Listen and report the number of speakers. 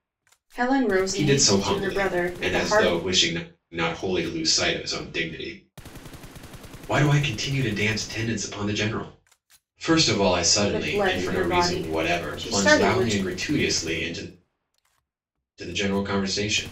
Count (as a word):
two